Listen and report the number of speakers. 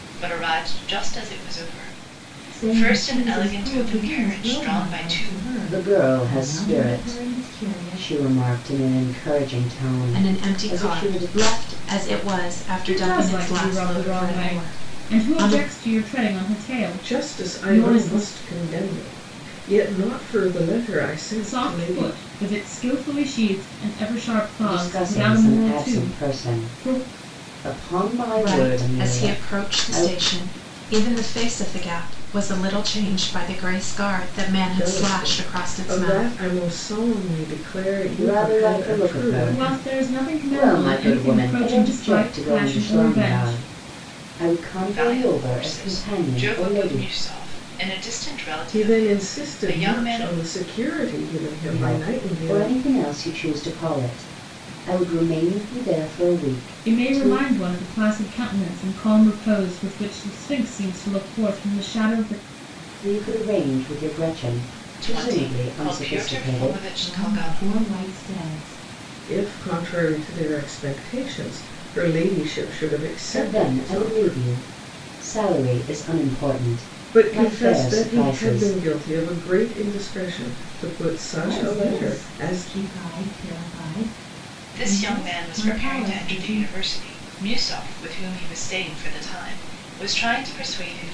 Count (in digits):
6